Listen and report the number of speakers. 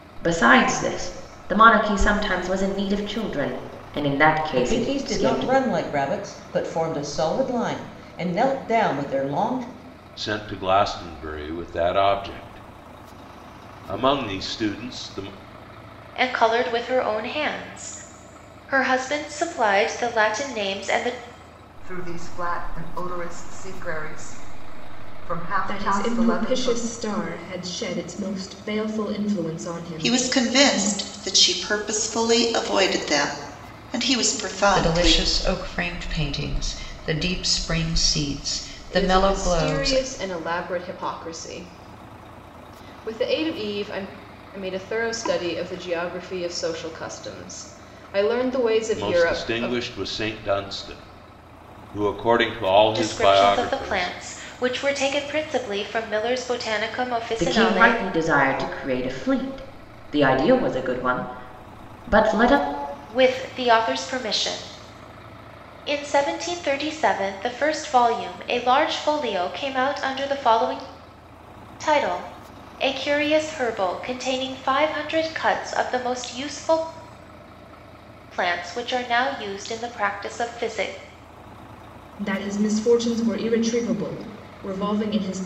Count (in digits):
9